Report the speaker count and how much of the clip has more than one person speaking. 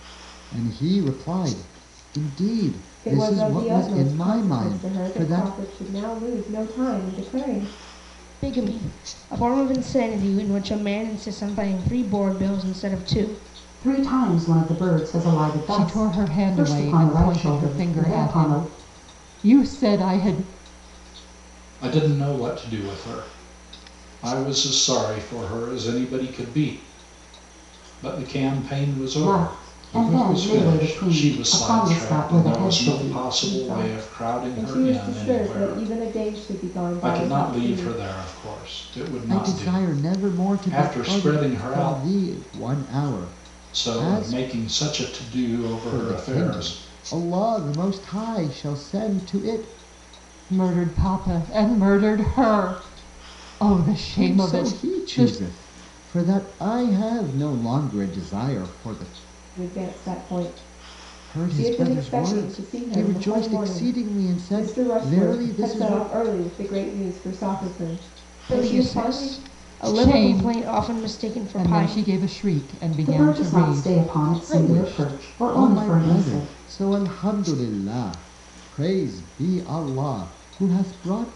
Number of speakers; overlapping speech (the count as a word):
six, about 36%